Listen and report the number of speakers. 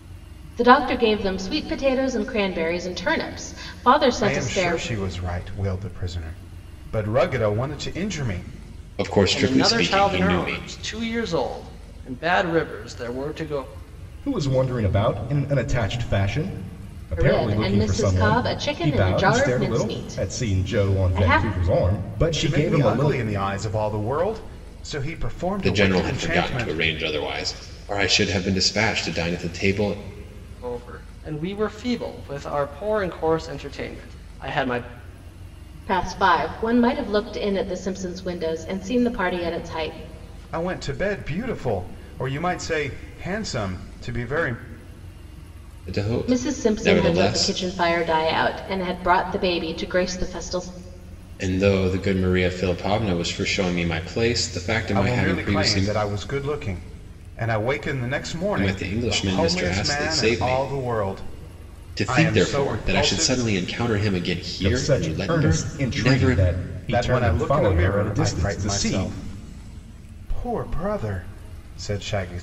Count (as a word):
five